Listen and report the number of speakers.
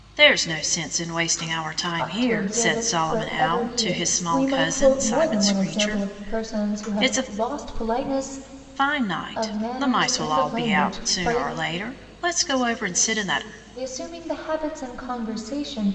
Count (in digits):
2